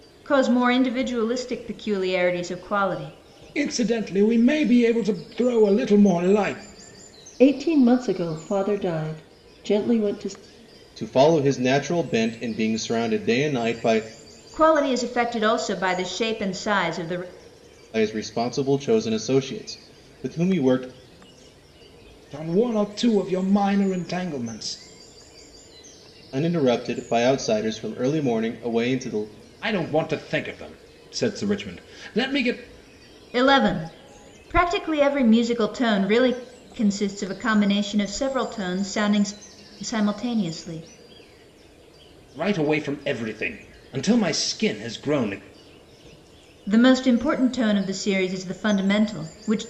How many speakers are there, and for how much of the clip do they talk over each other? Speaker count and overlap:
4, no overlap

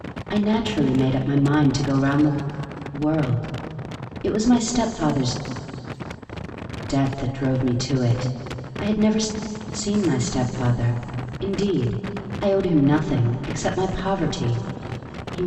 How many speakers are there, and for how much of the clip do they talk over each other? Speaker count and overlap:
1, no overlap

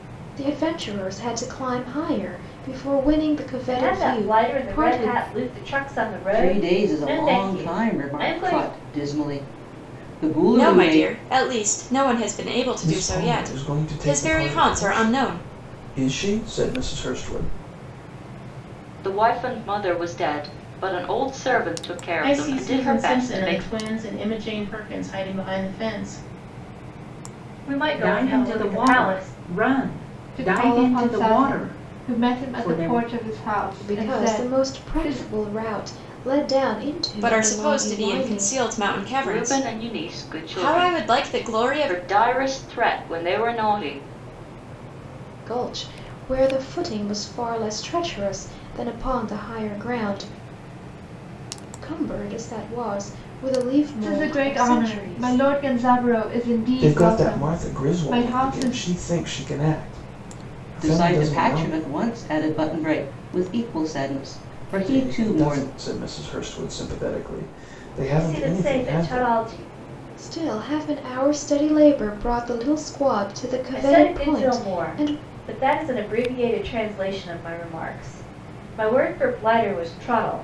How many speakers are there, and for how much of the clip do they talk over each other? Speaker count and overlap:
10, about 33%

